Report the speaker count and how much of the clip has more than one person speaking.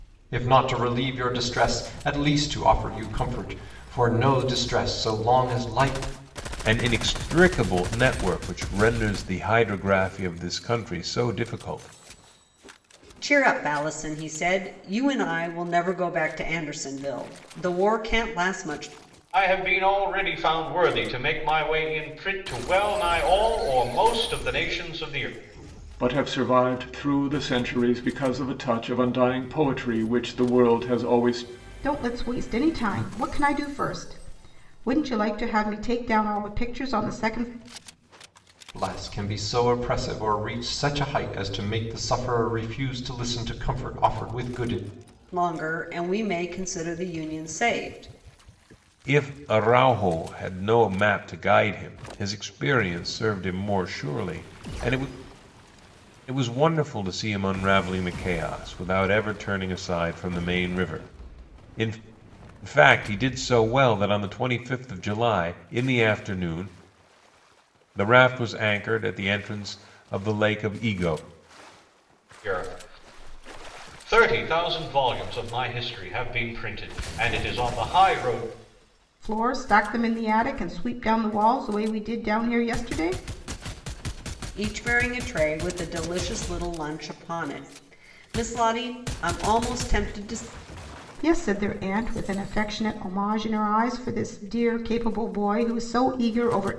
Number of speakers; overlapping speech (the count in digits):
6, no overlap